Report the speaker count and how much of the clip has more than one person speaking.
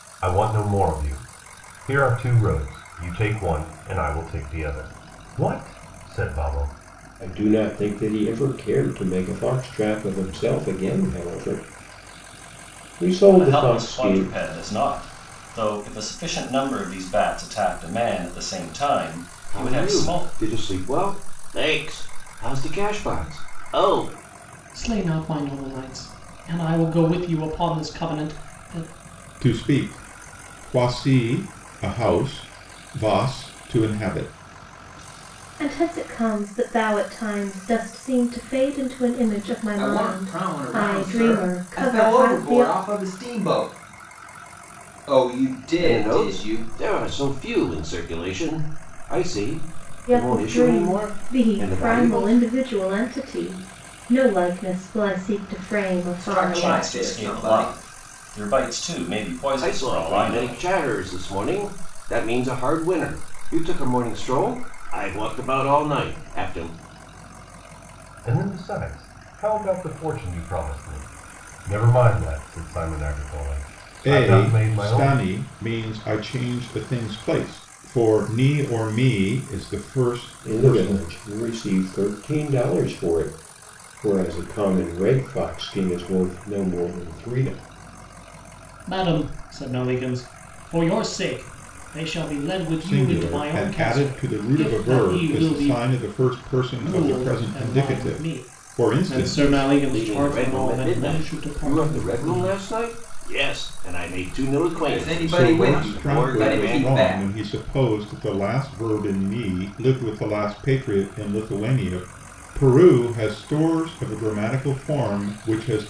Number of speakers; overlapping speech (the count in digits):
8, about 20%